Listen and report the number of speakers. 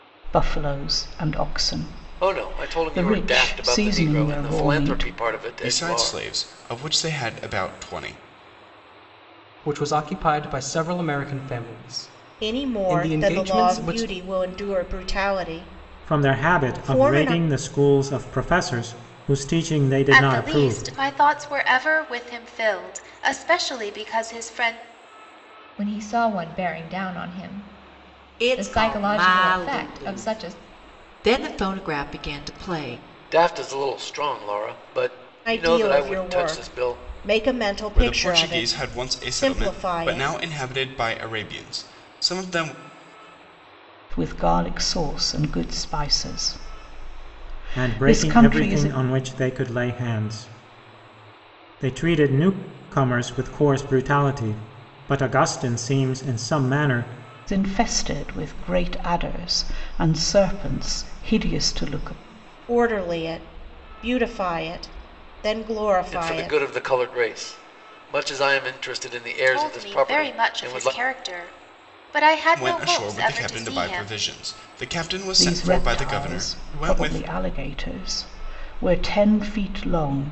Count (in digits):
9